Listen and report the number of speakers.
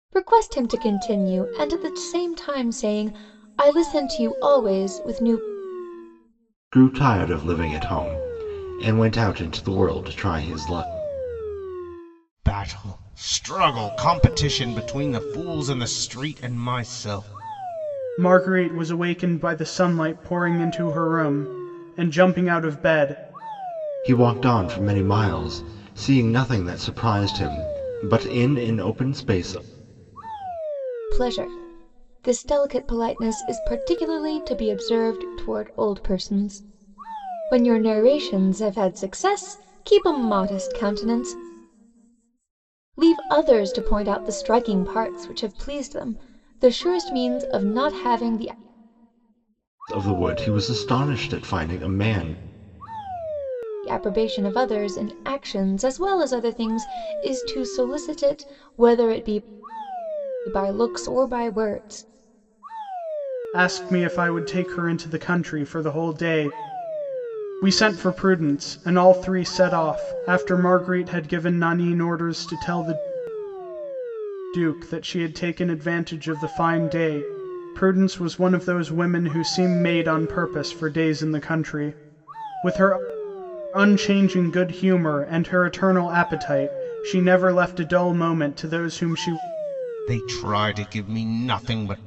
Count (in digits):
4